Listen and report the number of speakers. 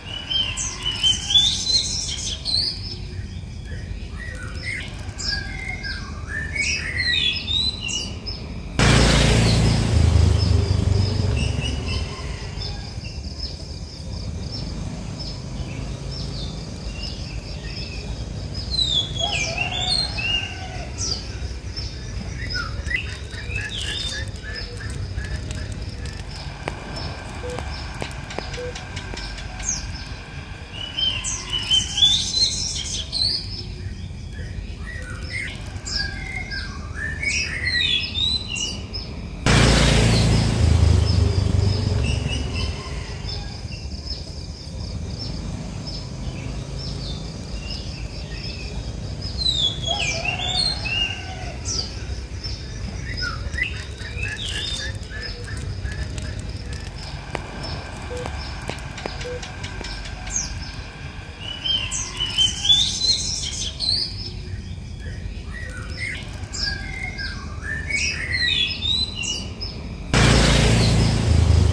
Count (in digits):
0